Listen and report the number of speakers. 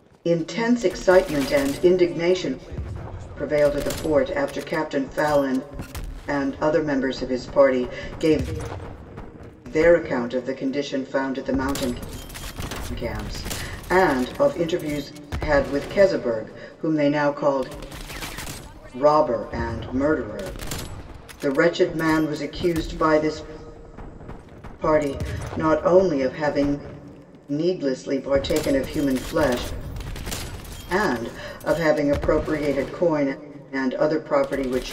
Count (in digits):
1